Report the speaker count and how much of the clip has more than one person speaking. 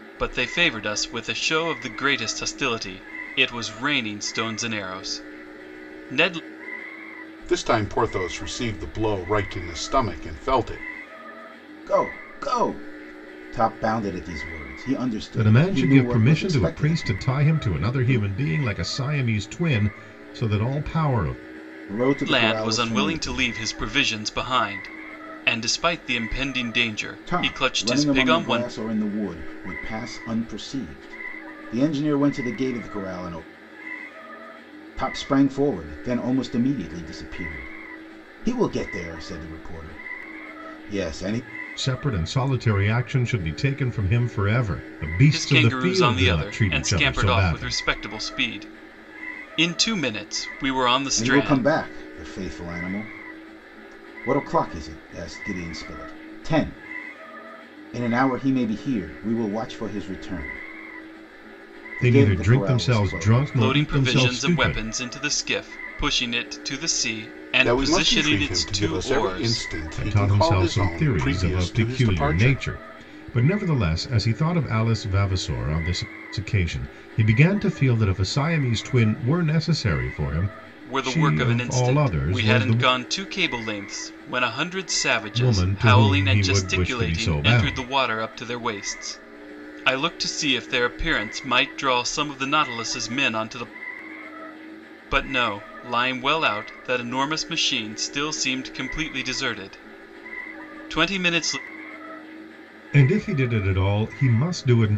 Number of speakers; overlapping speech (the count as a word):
four, about 20%